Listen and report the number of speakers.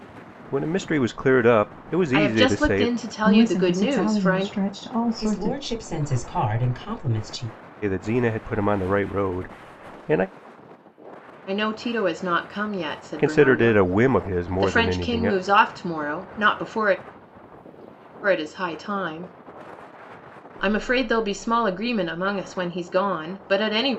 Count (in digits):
4